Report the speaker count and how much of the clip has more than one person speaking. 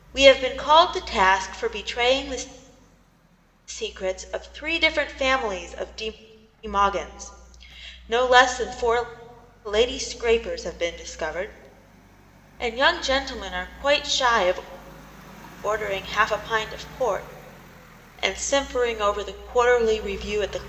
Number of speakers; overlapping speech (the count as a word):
one, no overlap